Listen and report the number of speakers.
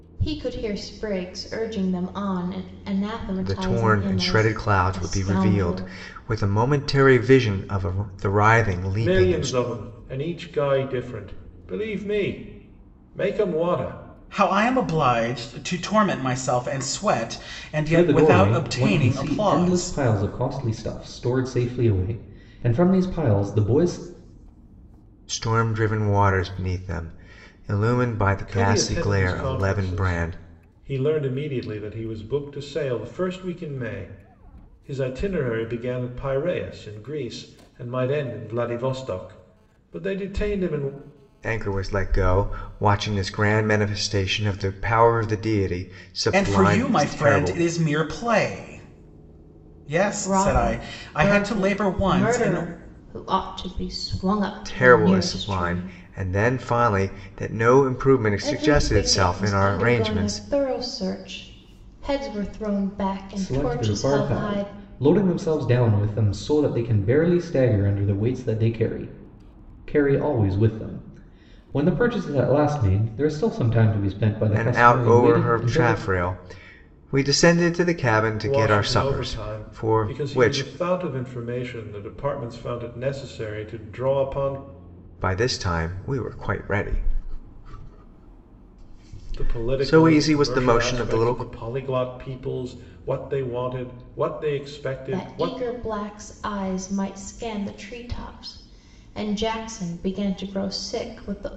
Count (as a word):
five